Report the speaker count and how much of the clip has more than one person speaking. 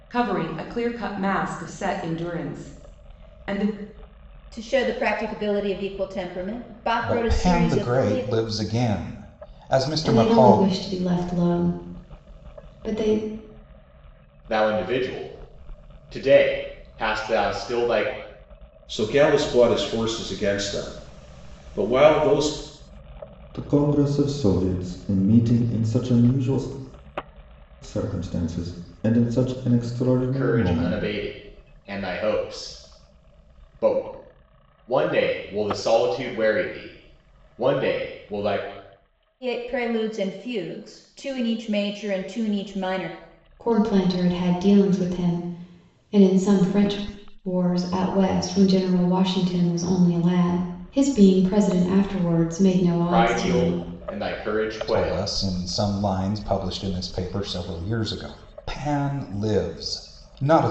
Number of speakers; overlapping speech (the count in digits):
7, about 7%